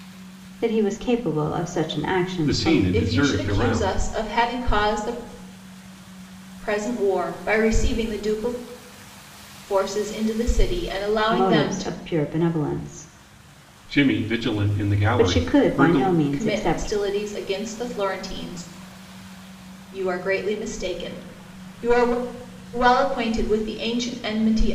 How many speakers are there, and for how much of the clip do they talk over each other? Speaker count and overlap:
3, about 16%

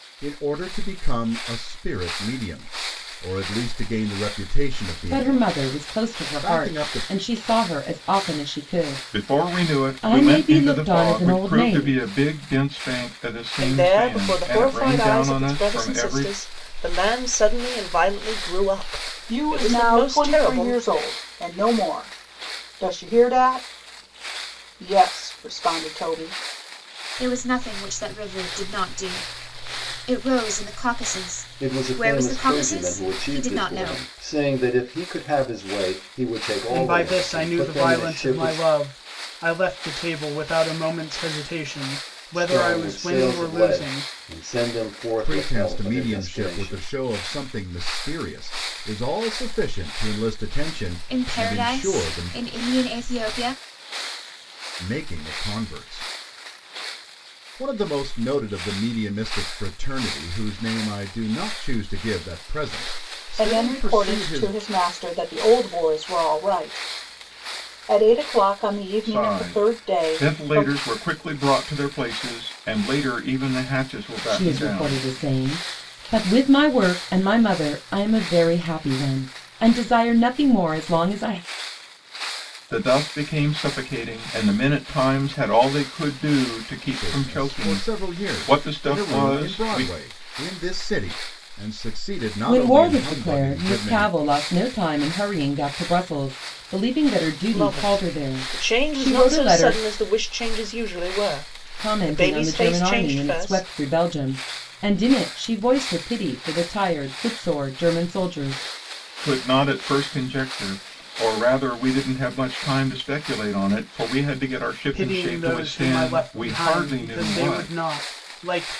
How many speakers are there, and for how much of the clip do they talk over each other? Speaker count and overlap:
8, about 29%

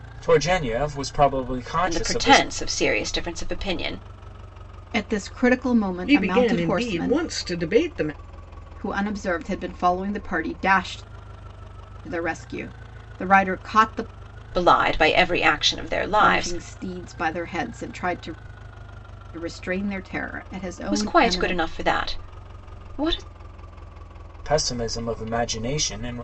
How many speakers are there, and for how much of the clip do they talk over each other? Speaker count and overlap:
4, about 12%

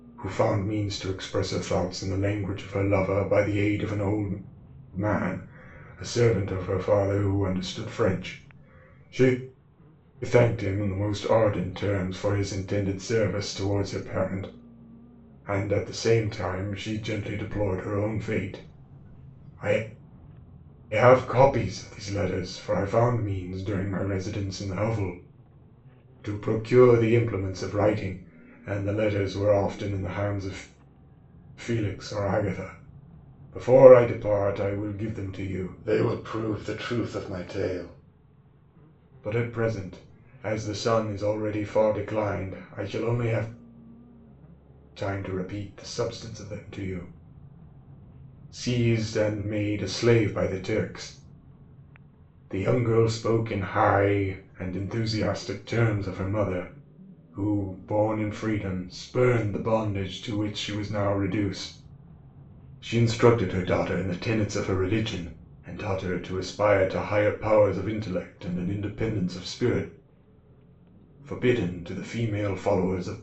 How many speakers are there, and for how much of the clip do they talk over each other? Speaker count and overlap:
1, no overlap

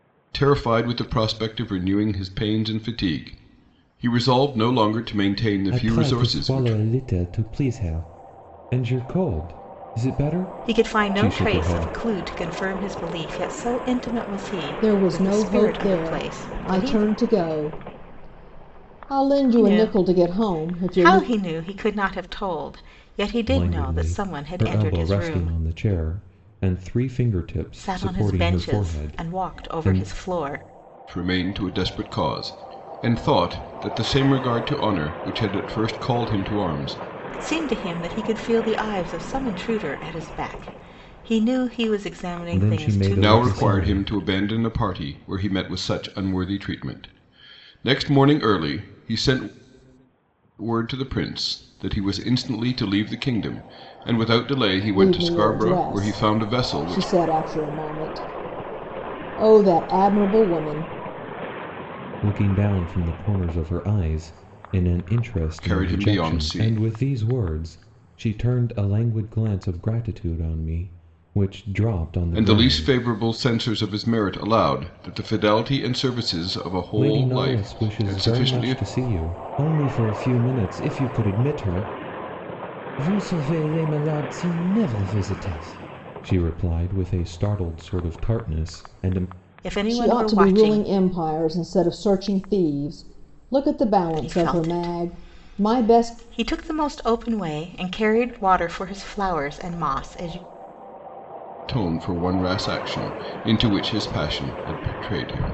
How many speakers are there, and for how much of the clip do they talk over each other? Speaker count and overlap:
4, about 20%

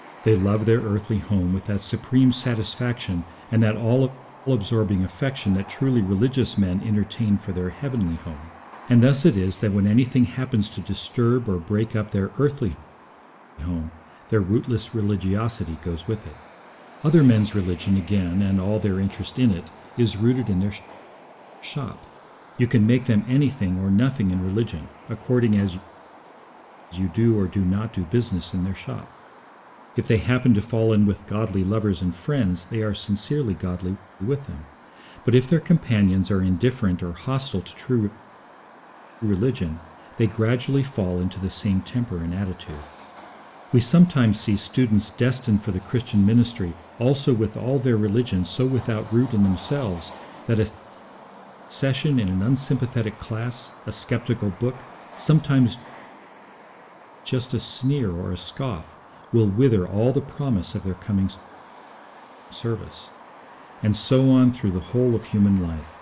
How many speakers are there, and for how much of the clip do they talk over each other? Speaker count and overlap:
1, no overlap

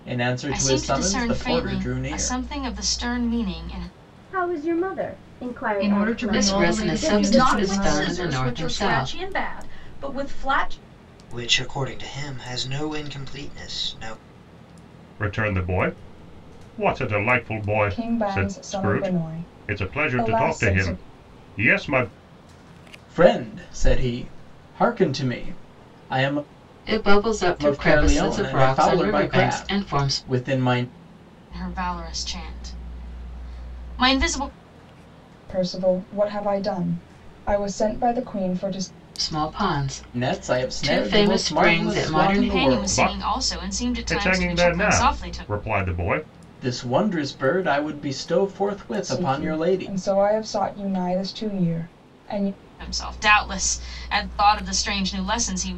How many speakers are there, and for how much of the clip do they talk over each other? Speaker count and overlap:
9, about 31%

